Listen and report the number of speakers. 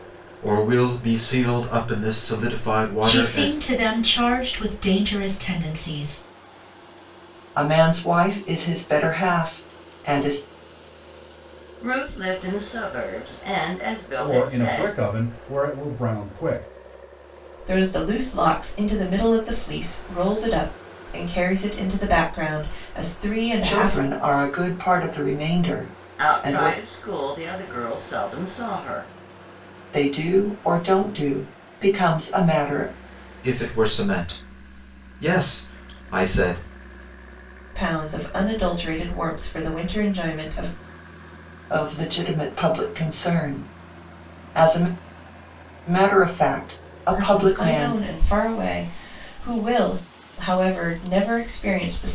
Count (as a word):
six